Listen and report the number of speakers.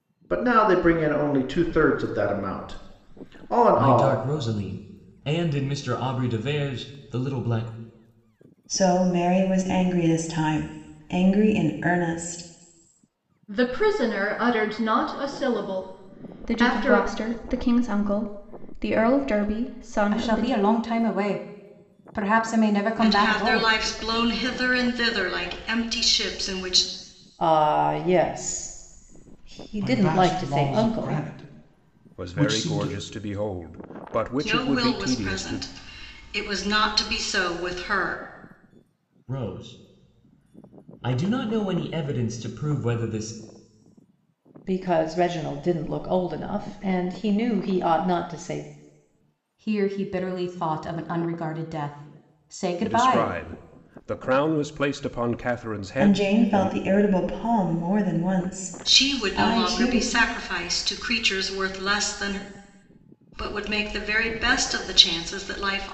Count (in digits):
10